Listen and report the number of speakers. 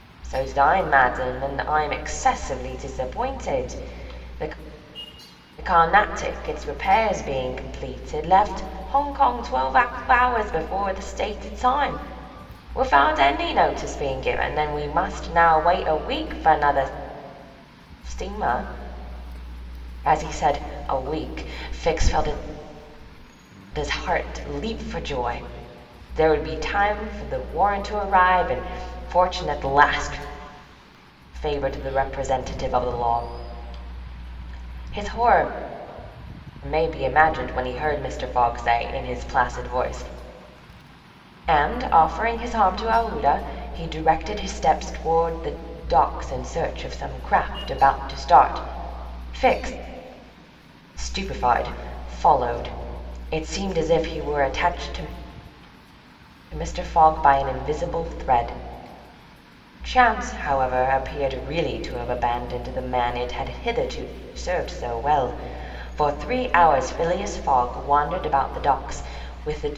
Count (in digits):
1